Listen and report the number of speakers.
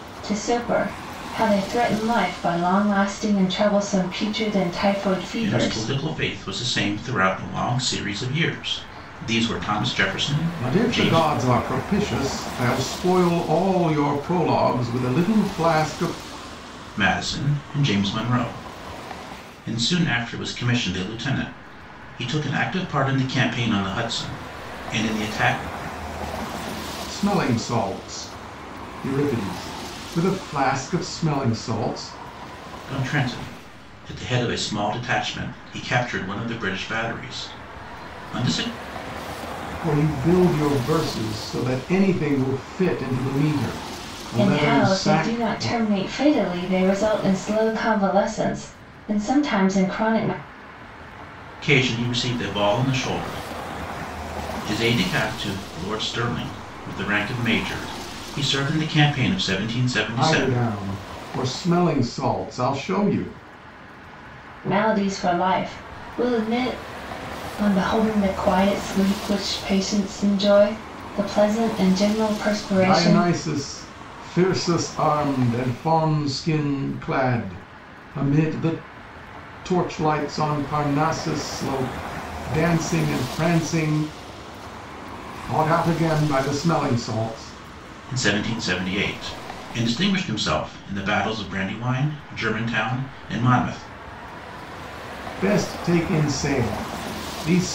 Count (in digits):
3